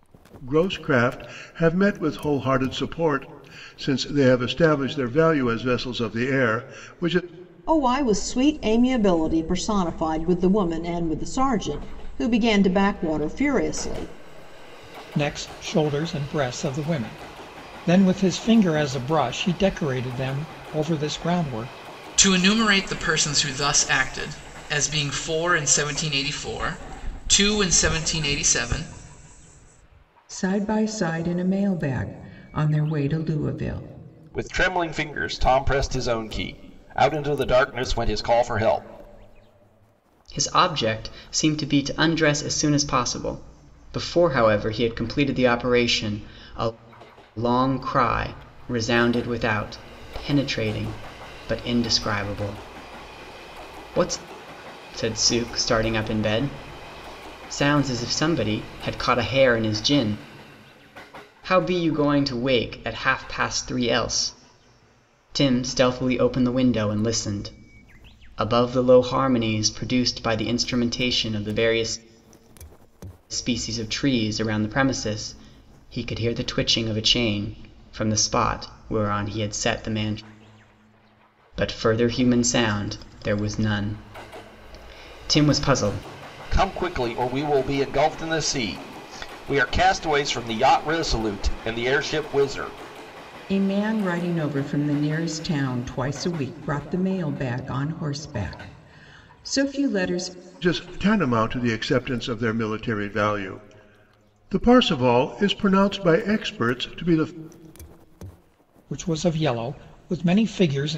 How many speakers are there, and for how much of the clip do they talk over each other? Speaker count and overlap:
seven, no overlap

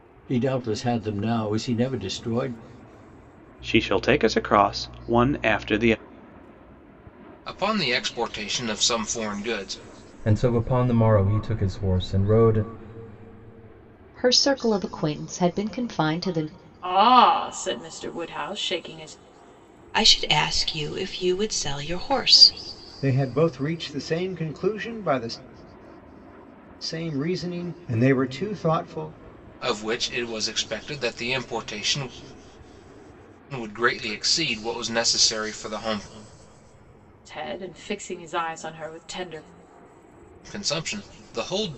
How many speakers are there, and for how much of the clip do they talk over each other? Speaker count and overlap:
eight, no overlap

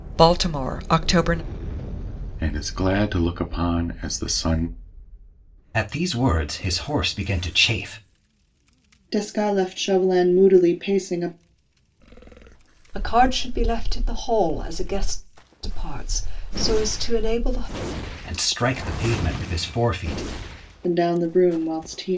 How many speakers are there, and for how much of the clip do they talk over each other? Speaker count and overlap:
five, no overlap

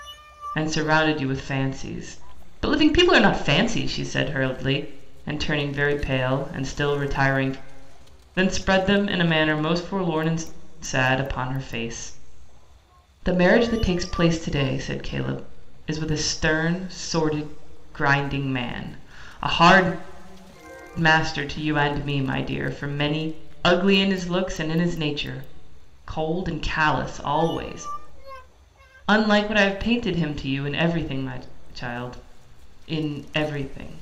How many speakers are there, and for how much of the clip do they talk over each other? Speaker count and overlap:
one, no overlap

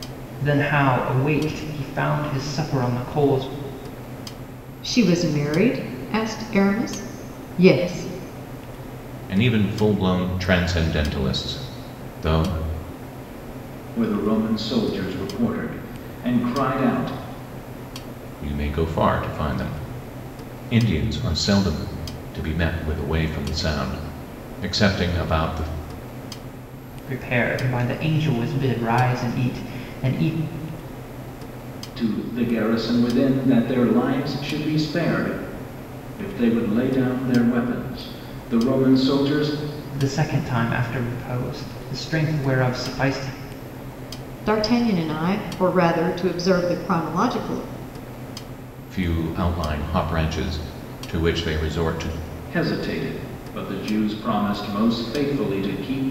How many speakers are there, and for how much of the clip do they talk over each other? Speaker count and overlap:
four, no overlap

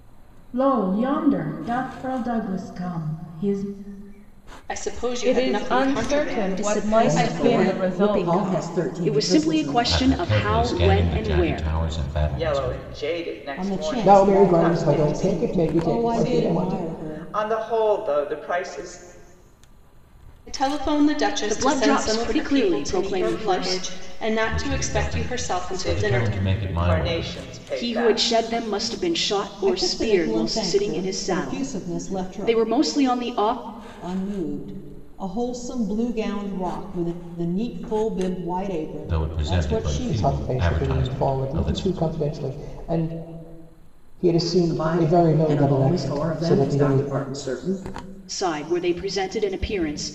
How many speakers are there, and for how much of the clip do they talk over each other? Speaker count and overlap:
ten, about 50%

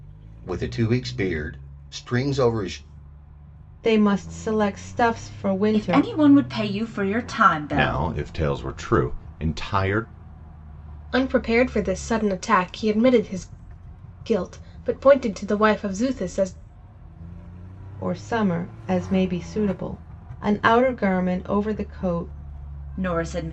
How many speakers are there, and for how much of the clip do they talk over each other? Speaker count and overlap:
five, about 3%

